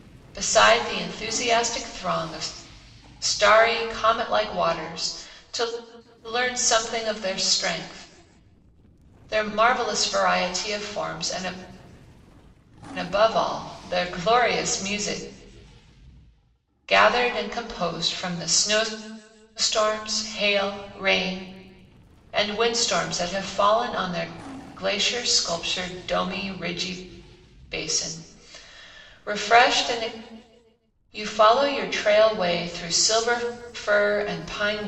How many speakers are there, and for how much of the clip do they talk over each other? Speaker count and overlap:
1, no overlap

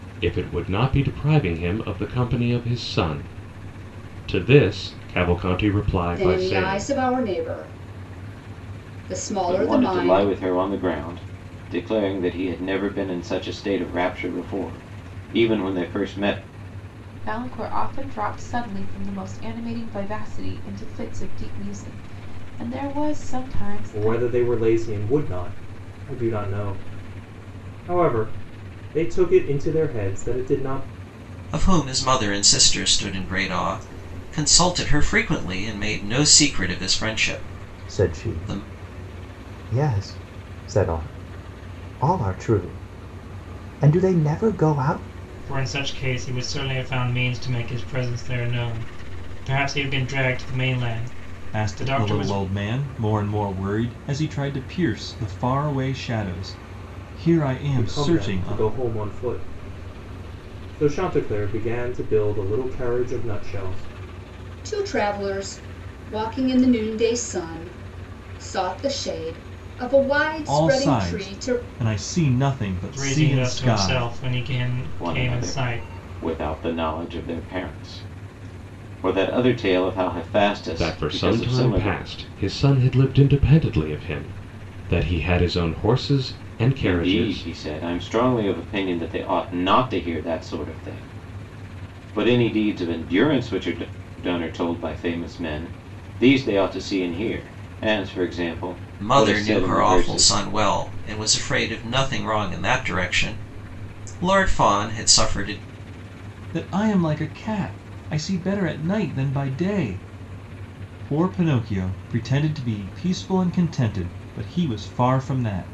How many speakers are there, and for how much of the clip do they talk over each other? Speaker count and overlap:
9, about 10%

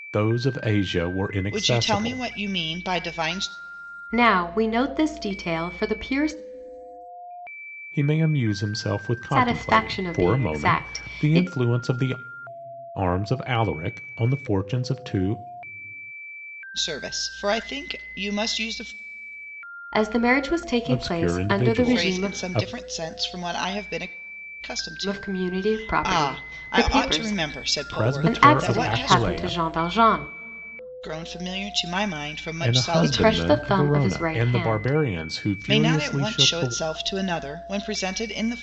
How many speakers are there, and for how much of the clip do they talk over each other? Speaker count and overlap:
3, about 33%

